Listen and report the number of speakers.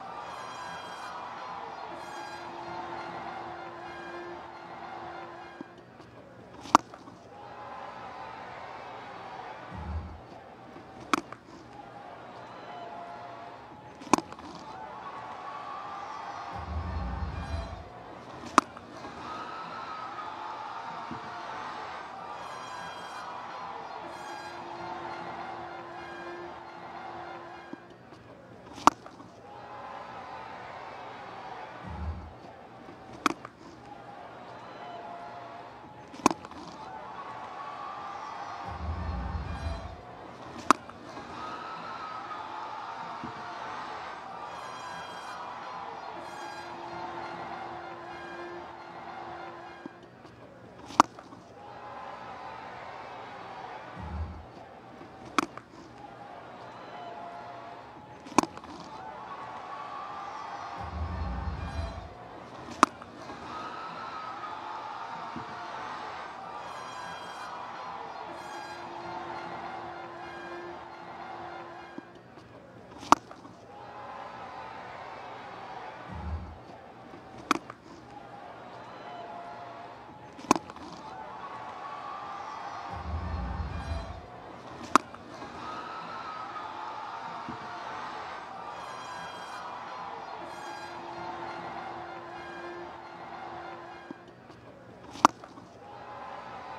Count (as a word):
zero